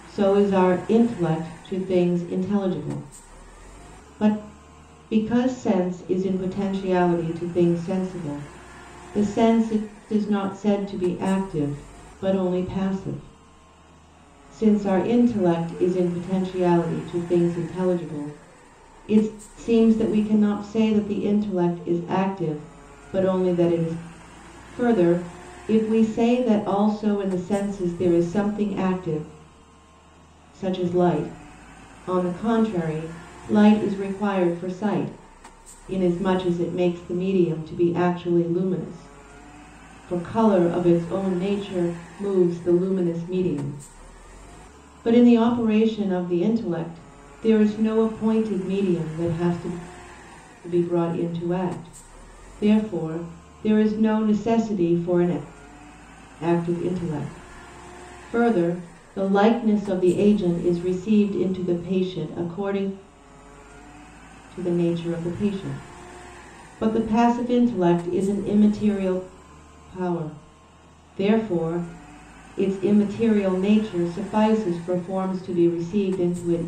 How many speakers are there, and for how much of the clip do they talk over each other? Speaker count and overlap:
1, no overlap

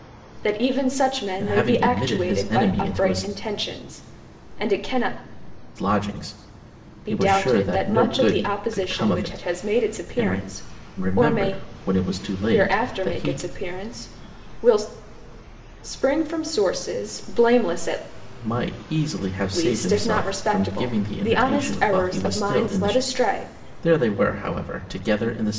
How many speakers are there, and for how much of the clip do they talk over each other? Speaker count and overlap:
2, about 40%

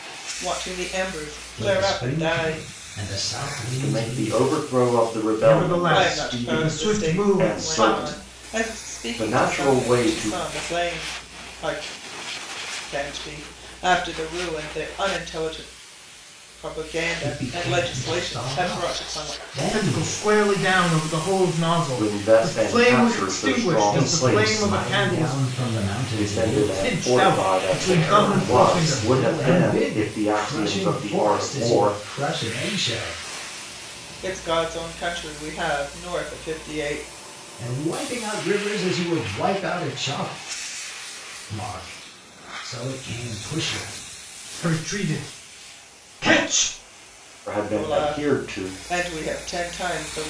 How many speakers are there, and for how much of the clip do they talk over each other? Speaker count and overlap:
4, about 39%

